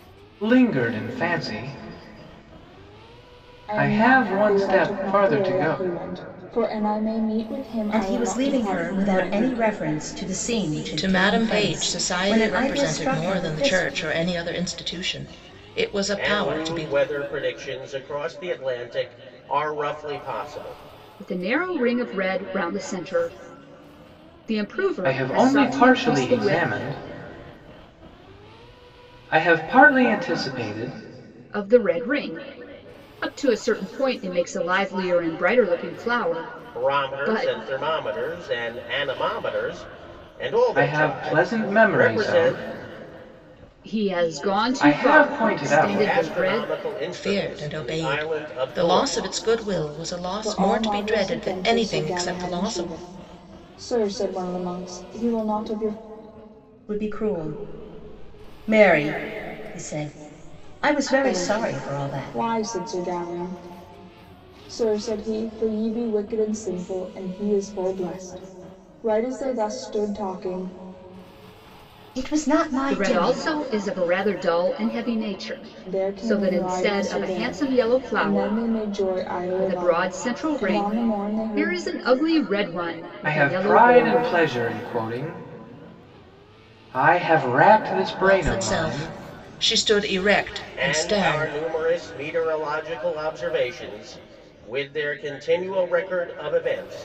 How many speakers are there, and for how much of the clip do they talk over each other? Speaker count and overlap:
six, about 30%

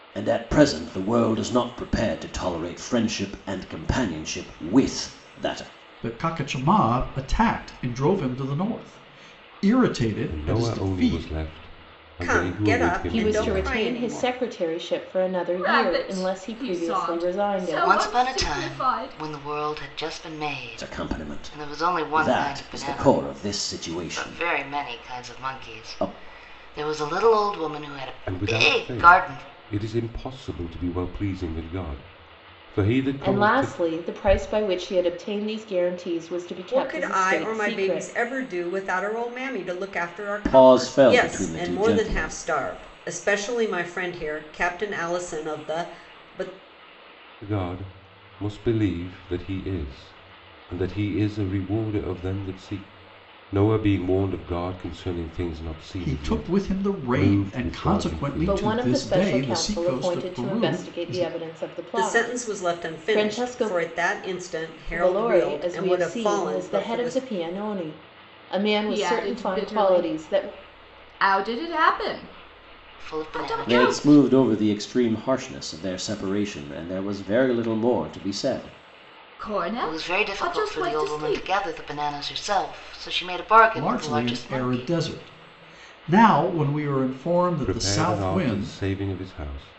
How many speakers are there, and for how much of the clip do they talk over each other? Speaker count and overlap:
seven, about 37%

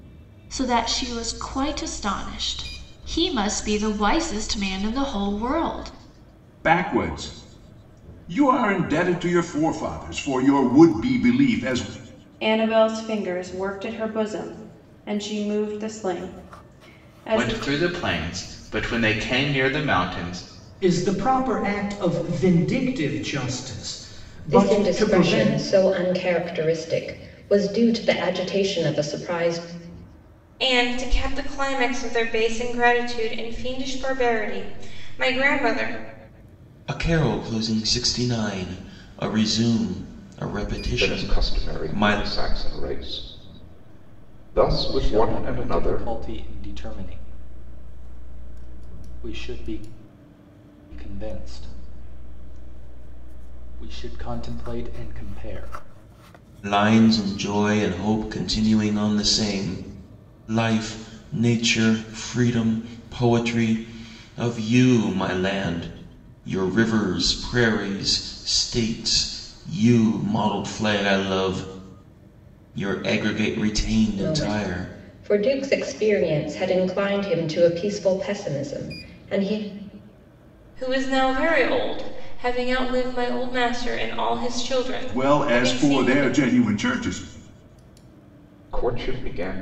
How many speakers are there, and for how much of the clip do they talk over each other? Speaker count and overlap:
ten, about 7%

